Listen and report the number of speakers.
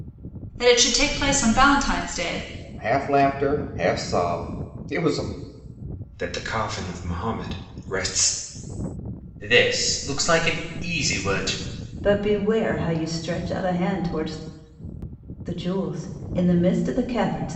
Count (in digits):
5